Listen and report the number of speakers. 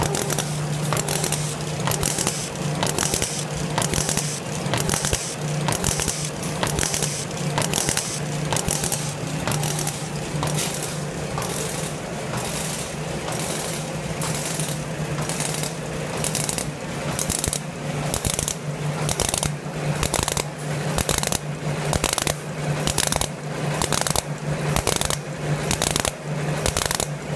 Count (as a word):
zero